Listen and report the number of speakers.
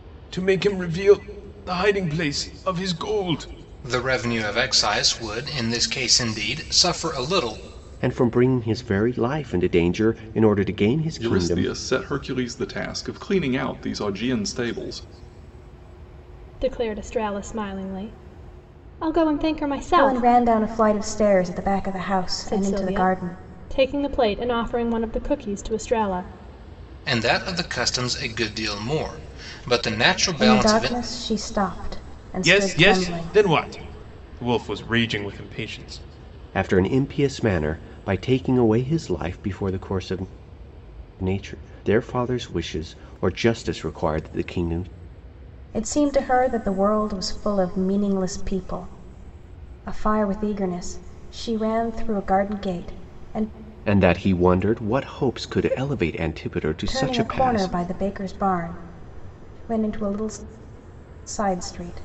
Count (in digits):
6